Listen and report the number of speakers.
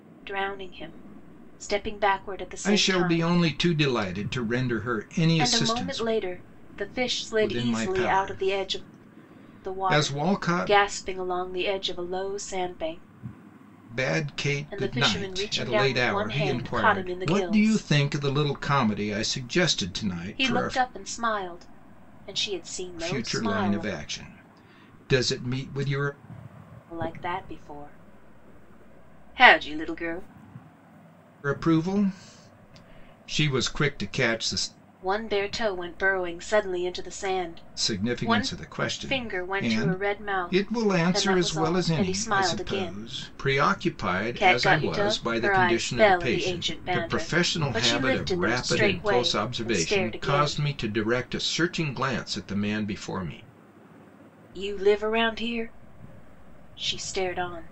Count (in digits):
2